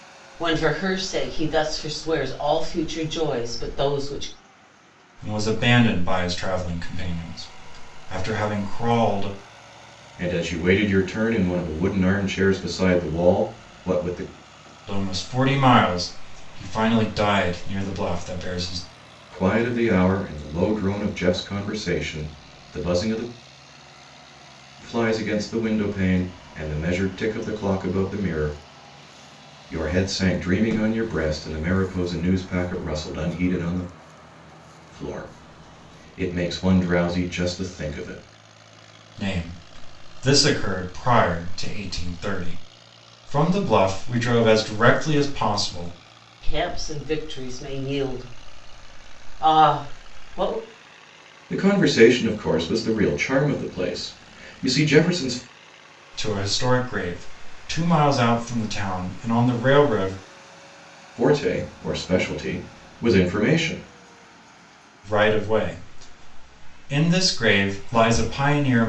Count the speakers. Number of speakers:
three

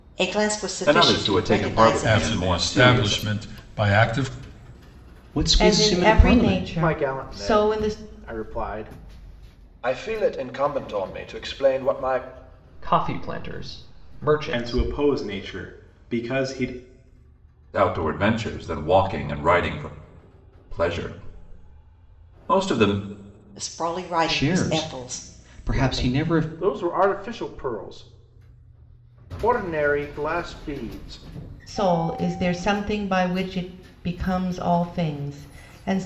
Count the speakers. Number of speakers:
nine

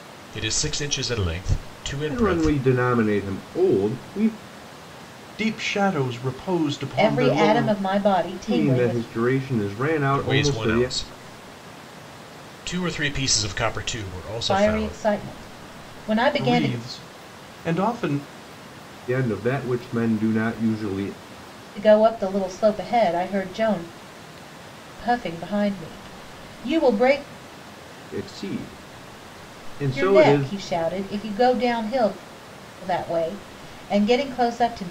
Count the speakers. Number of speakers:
four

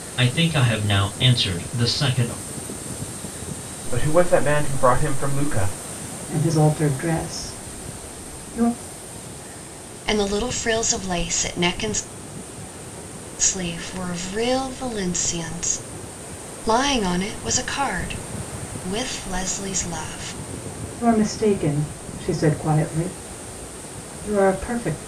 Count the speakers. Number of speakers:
four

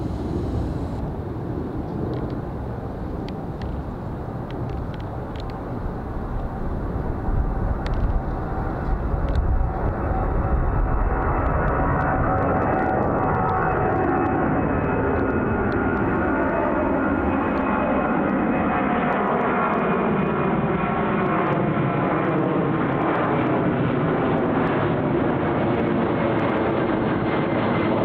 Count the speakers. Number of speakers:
zero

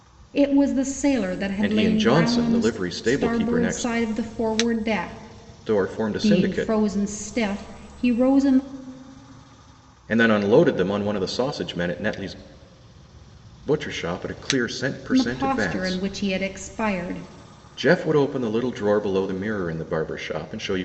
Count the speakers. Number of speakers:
two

